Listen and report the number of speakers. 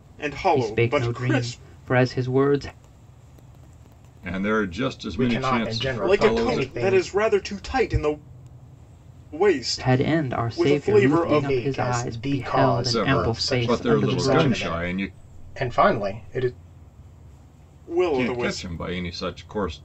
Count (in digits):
4